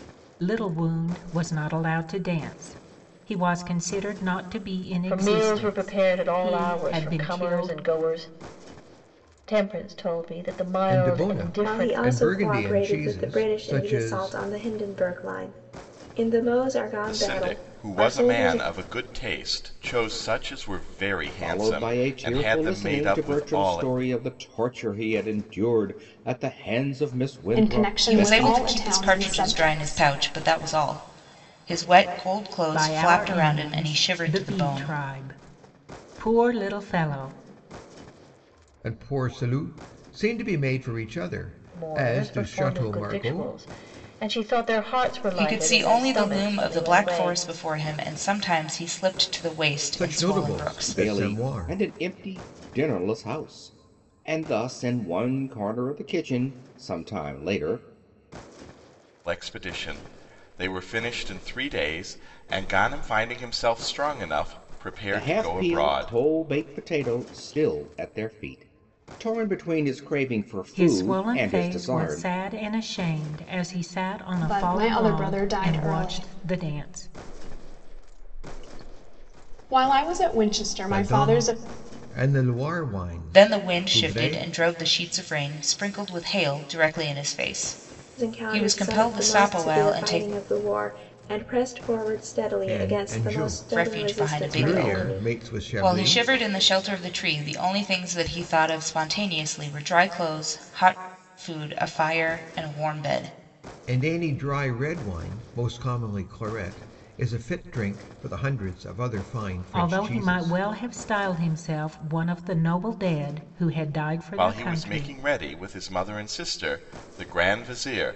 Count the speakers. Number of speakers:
8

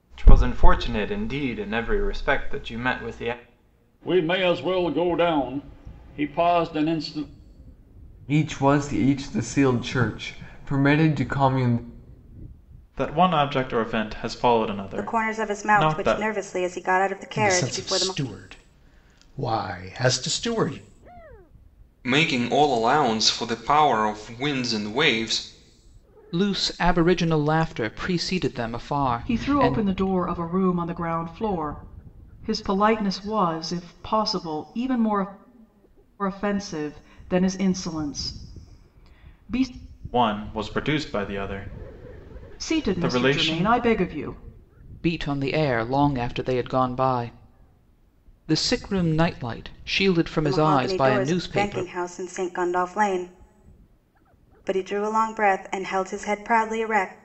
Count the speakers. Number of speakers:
9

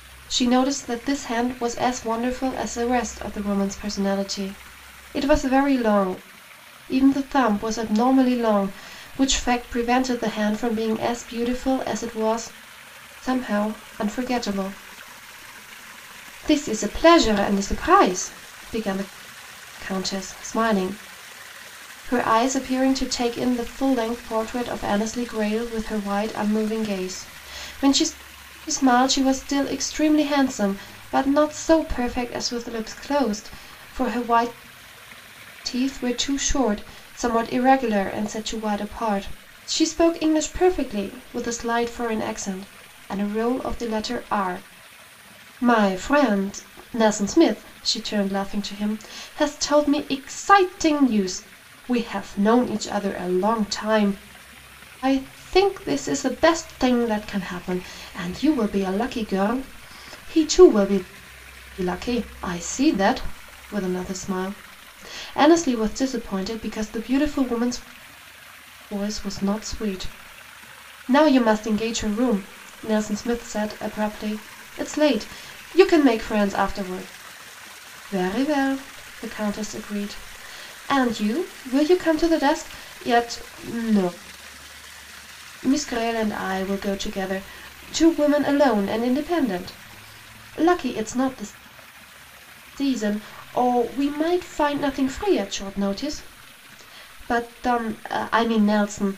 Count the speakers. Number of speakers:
1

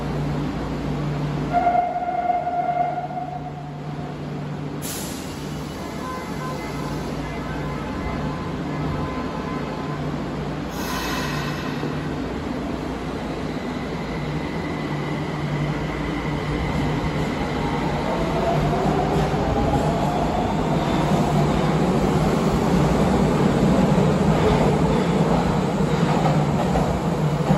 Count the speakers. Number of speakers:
0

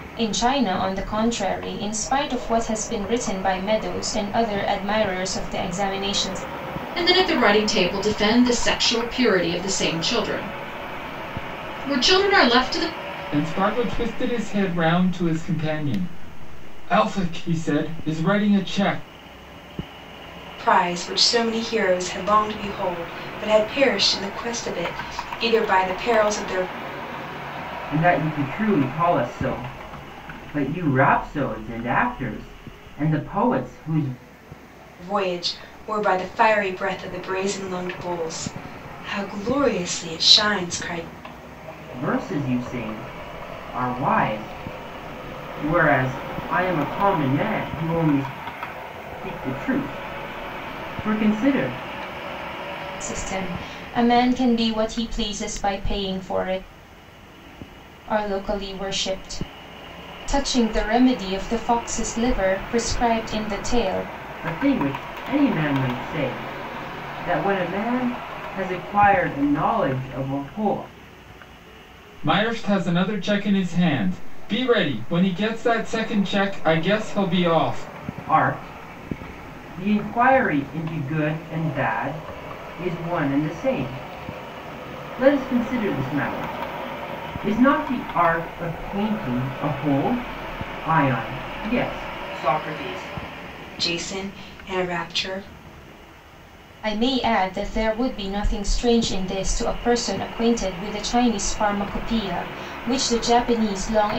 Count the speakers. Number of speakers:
5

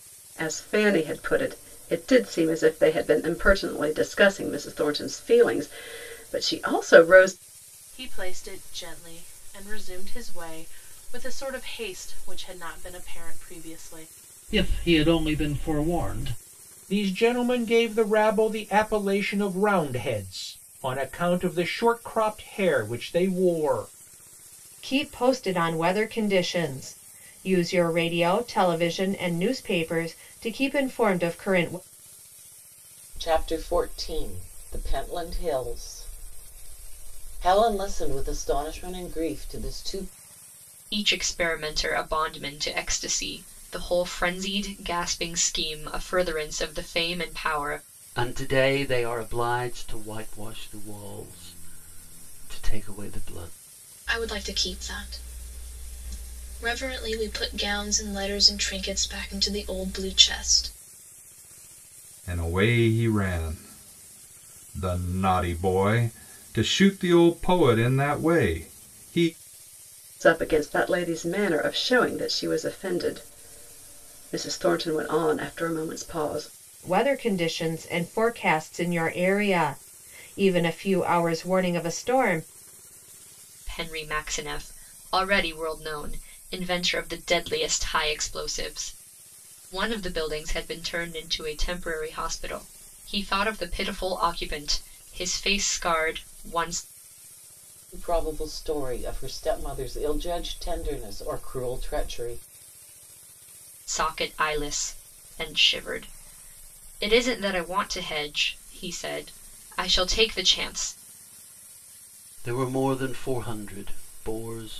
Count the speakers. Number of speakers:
10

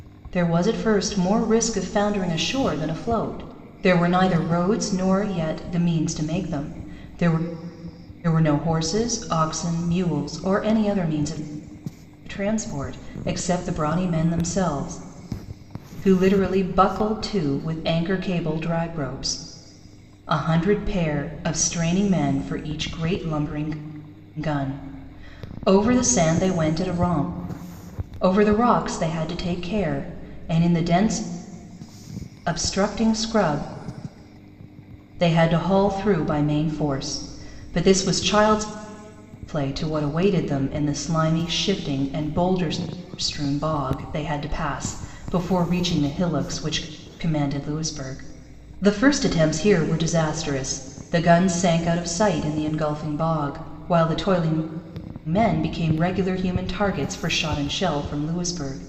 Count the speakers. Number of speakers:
1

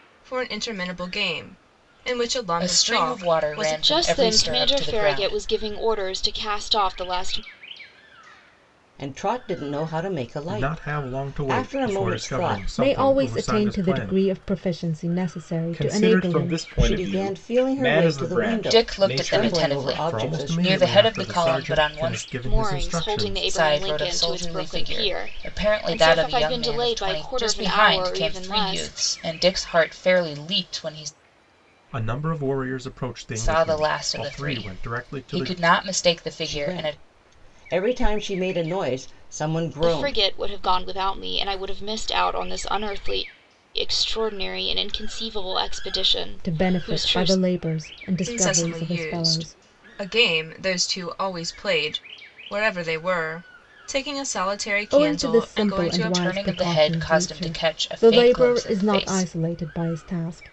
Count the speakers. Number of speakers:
7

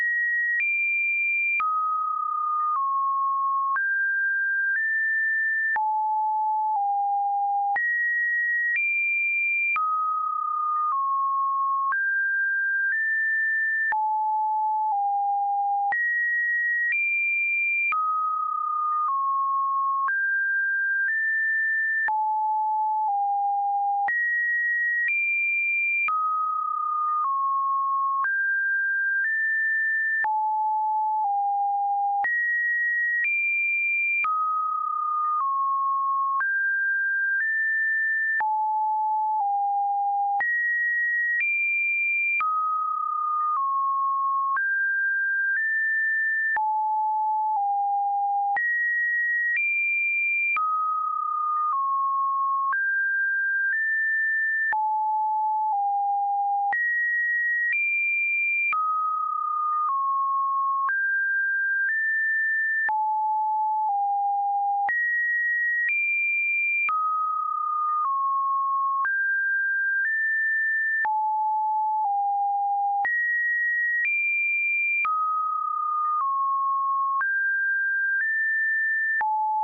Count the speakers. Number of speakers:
0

